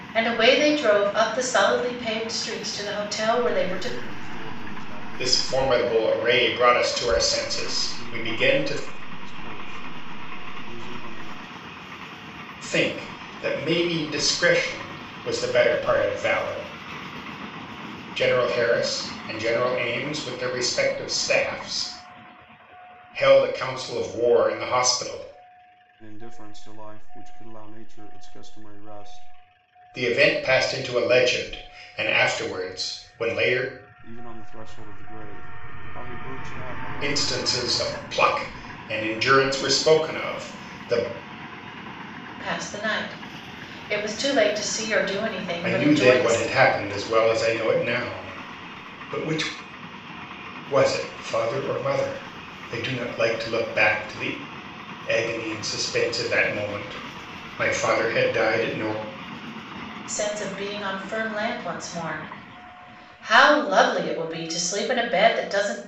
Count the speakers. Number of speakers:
3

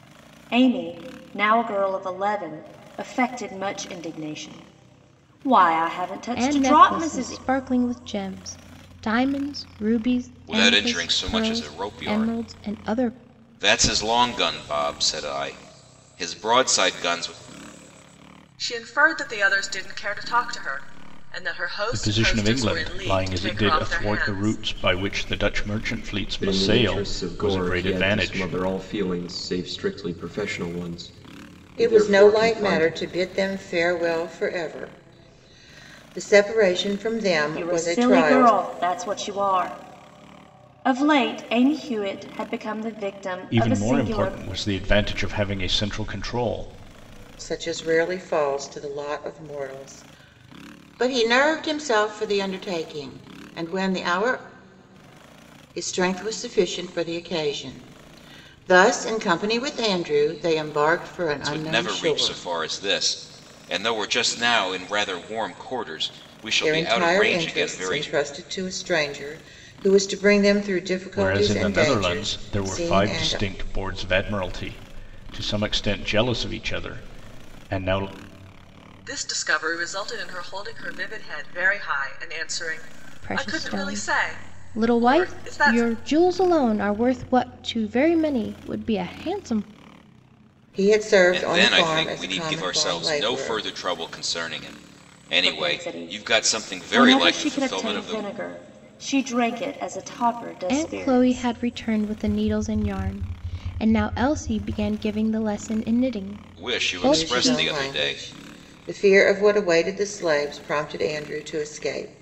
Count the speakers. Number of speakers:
7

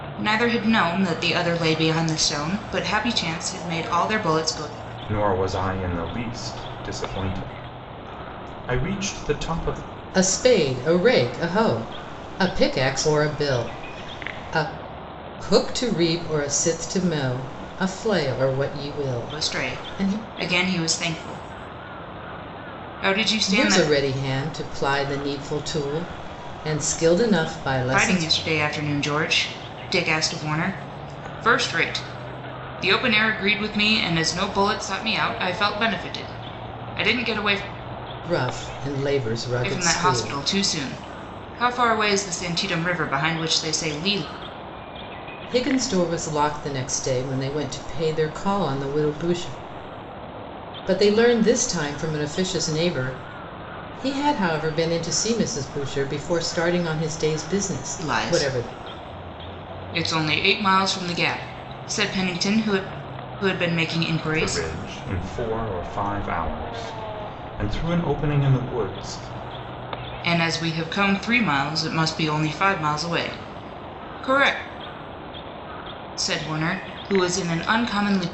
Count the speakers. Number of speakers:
3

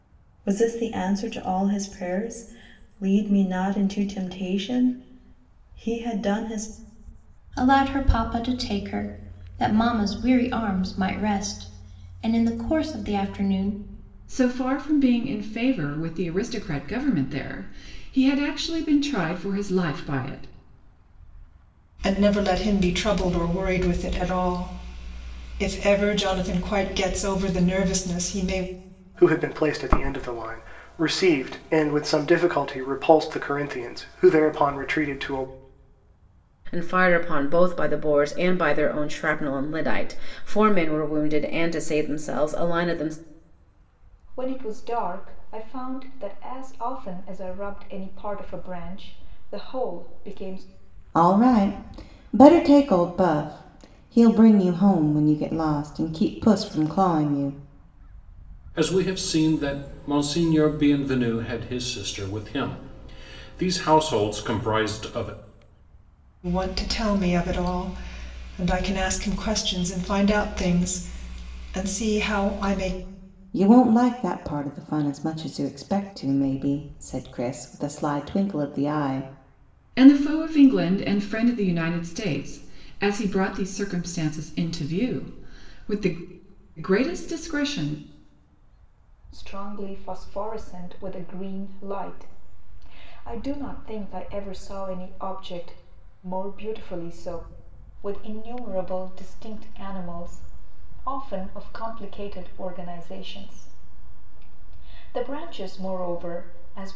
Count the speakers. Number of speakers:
9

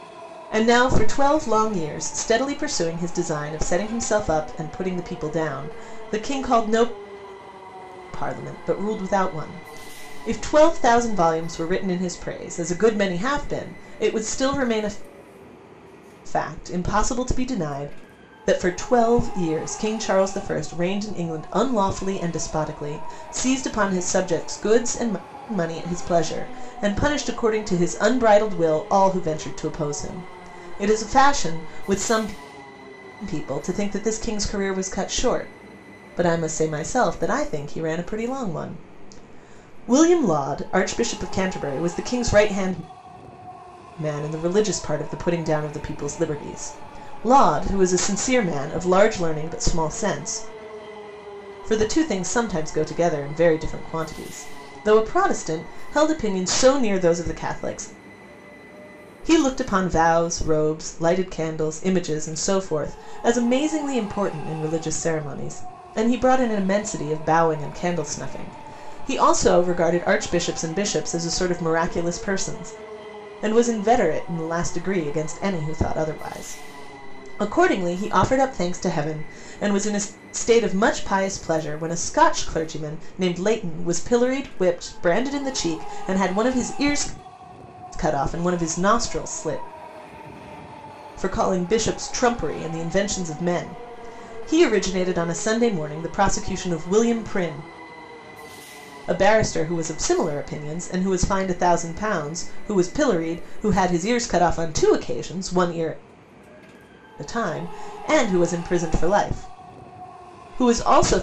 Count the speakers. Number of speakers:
1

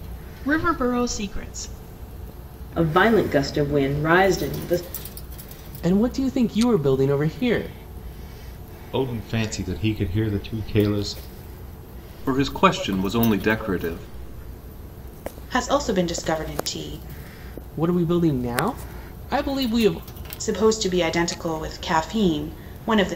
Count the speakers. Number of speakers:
6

